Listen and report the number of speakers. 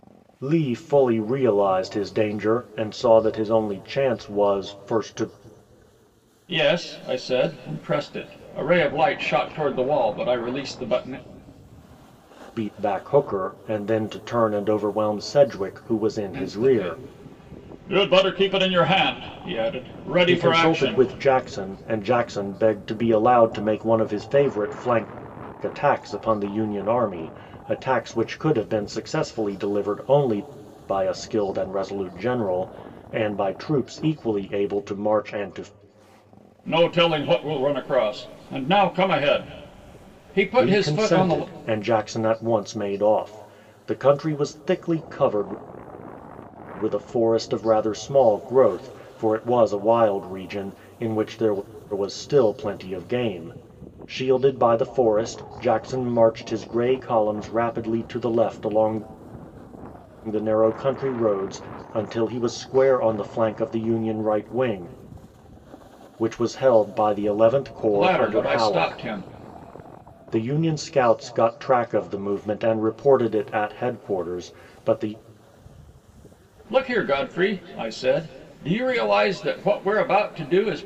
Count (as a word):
two